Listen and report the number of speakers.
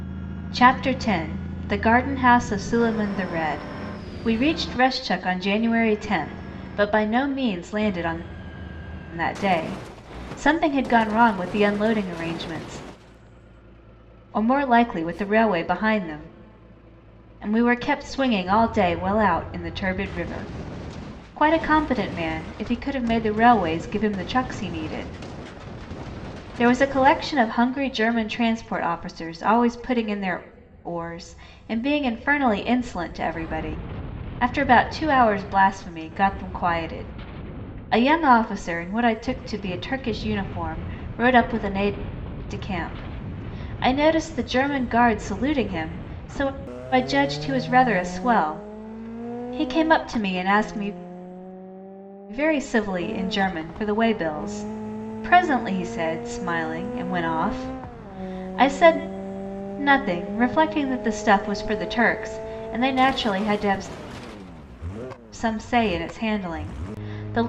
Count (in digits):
1